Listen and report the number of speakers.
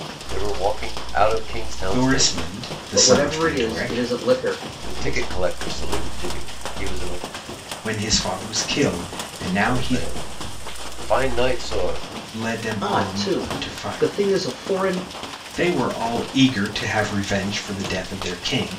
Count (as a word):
three